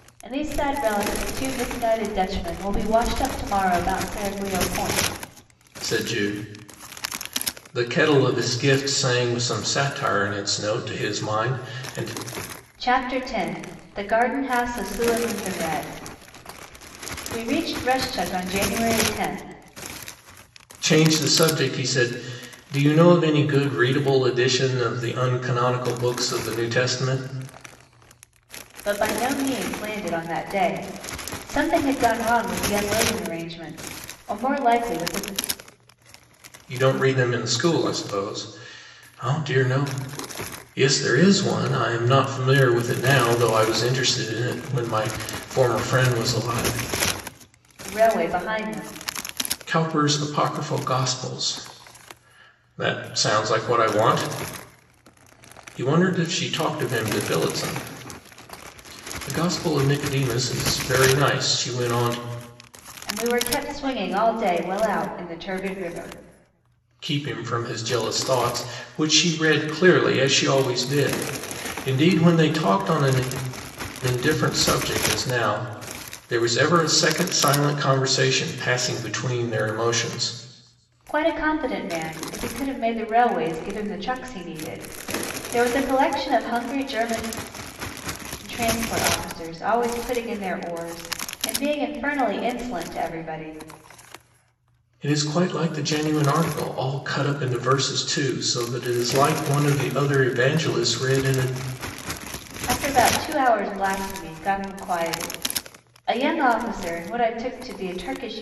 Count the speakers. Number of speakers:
2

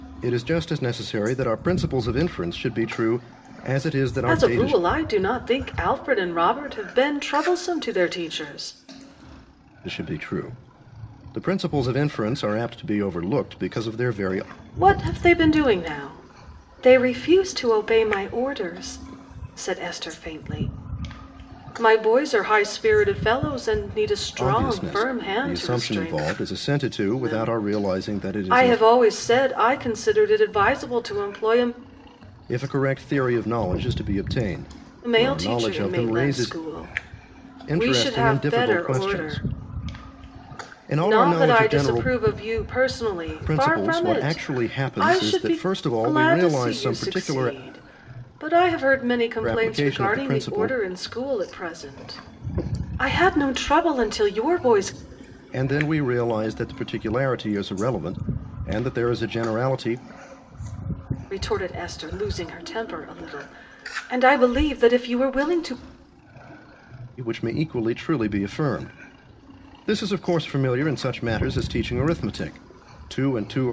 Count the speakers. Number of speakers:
2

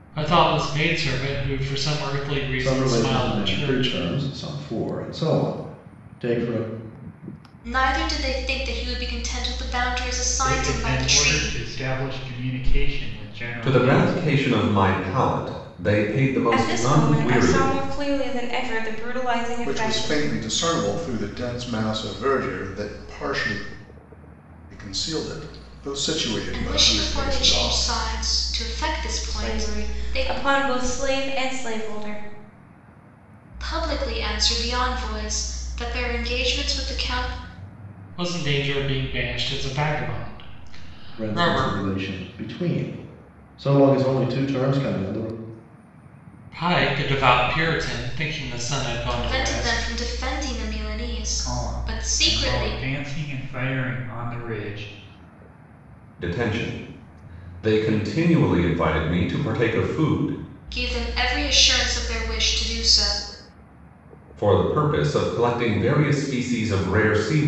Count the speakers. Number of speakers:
7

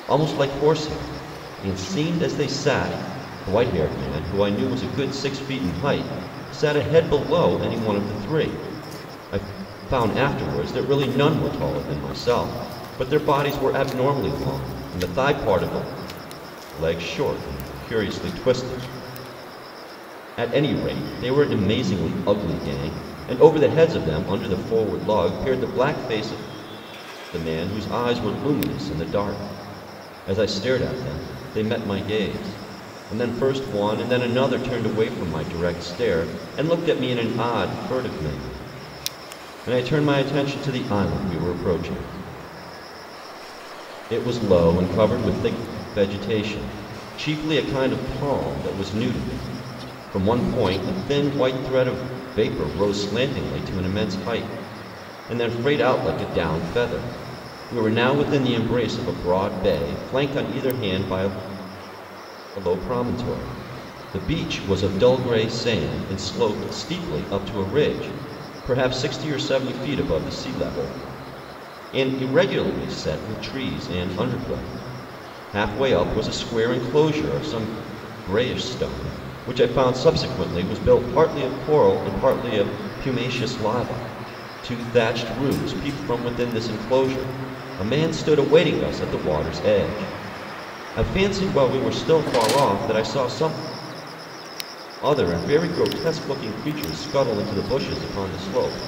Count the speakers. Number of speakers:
1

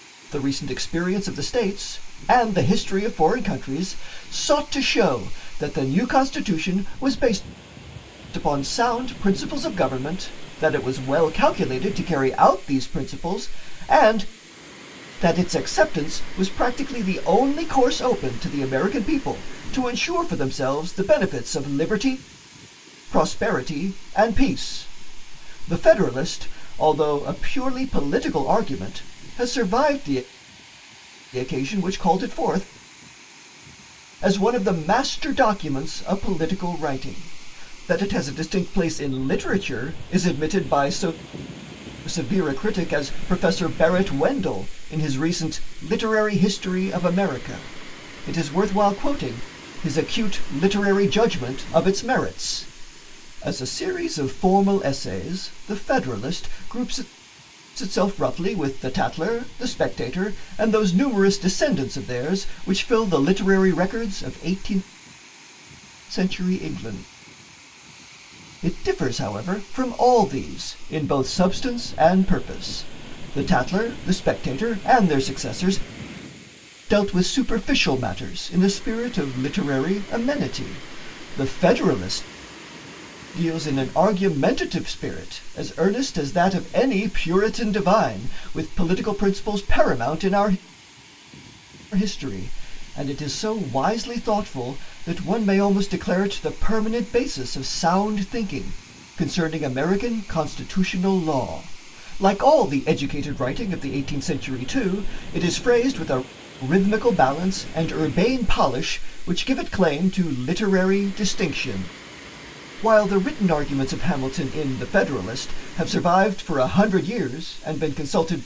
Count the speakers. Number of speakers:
1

